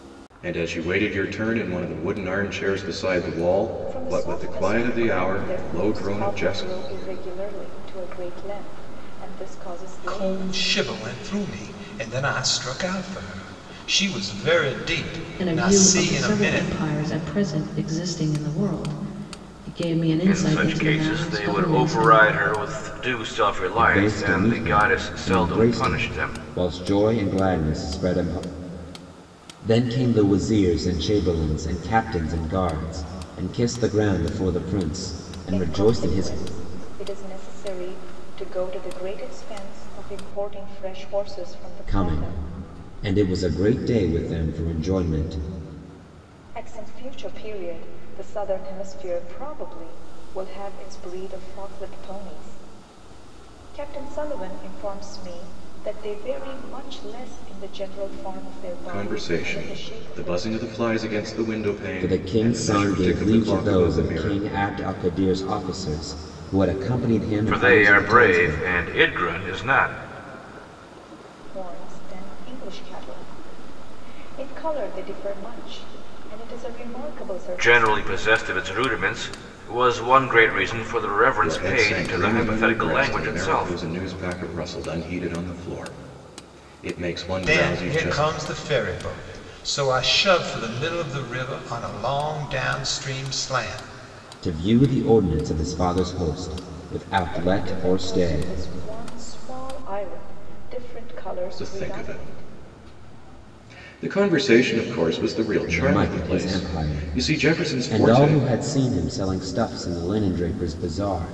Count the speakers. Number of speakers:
six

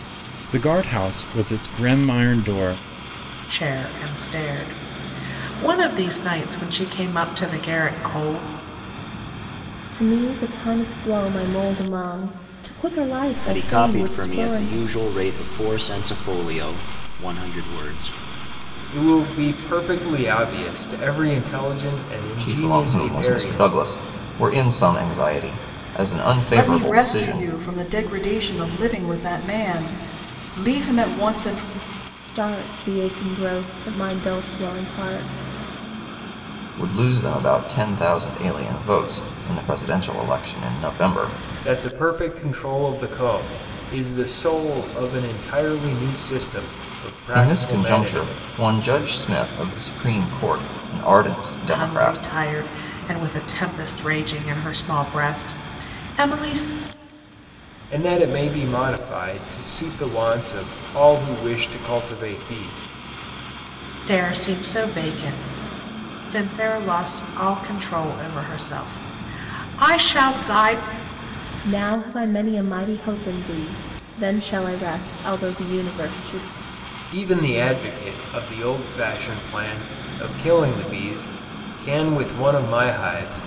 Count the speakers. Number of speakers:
seven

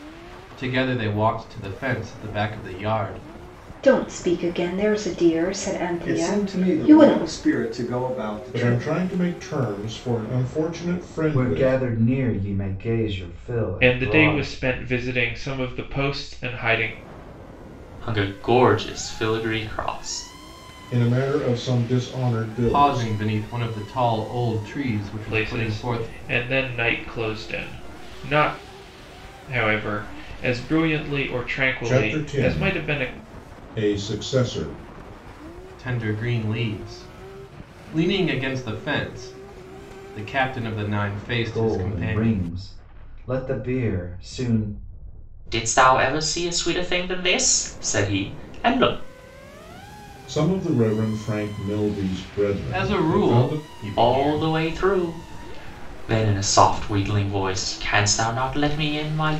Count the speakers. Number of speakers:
seven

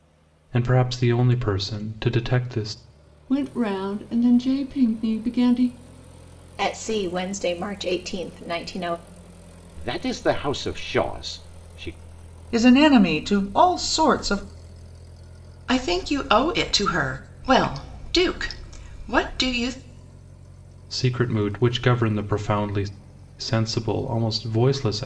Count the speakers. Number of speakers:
six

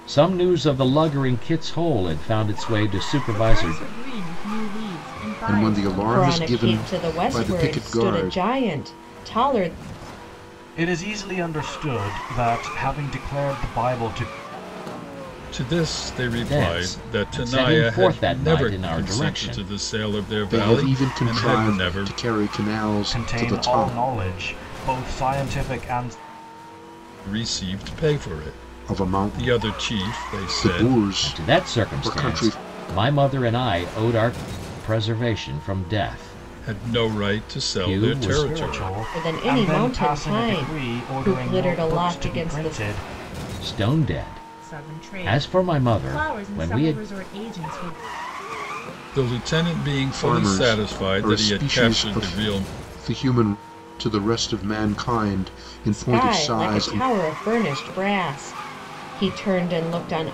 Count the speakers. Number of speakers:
seven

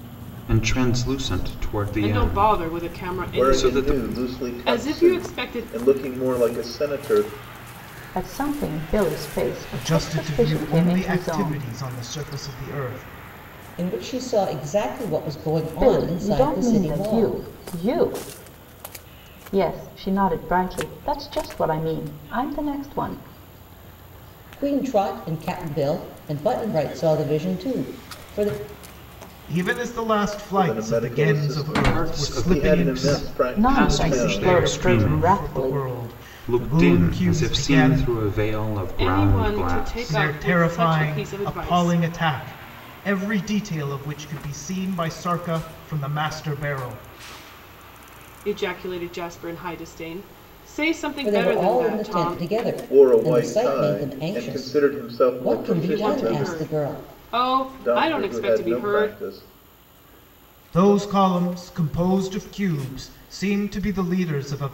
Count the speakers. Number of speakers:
six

